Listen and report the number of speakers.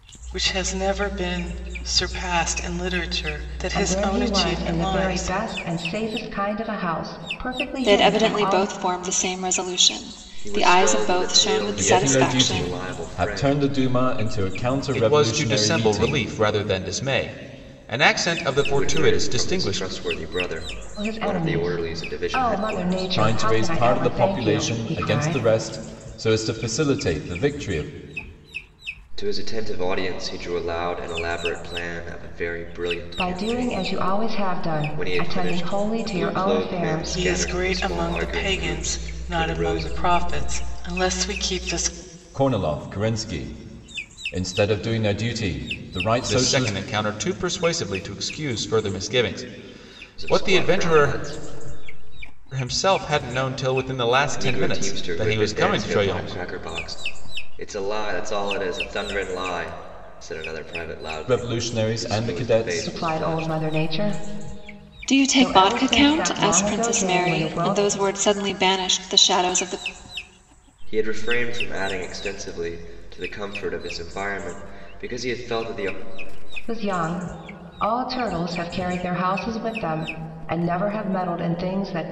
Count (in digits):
6